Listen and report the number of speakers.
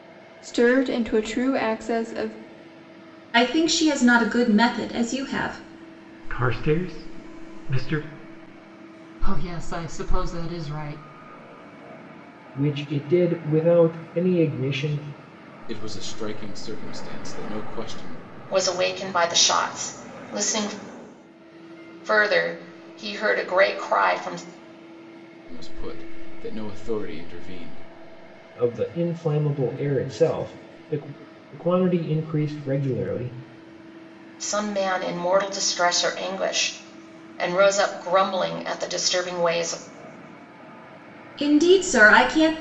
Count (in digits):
7